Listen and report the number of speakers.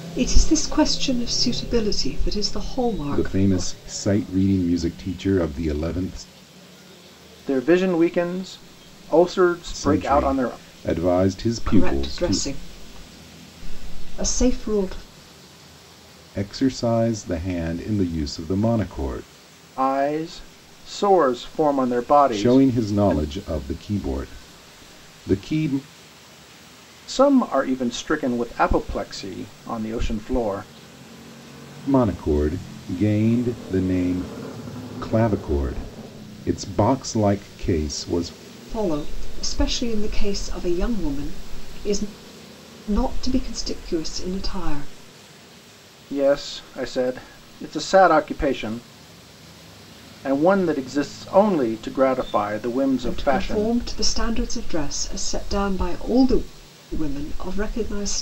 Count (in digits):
3